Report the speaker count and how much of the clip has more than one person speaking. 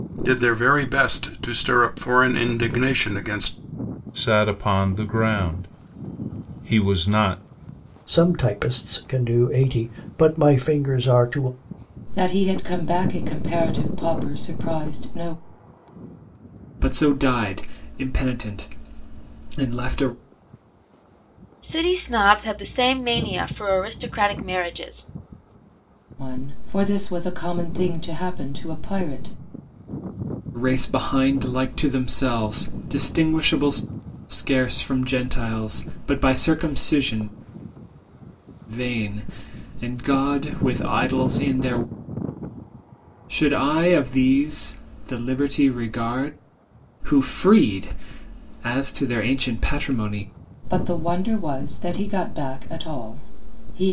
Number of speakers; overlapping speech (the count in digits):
6, no overlap